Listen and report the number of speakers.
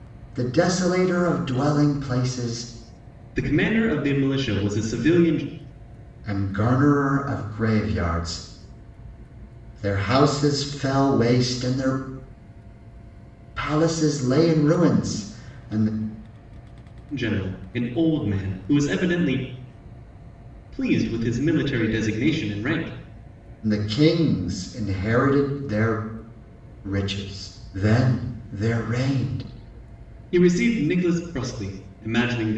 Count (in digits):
2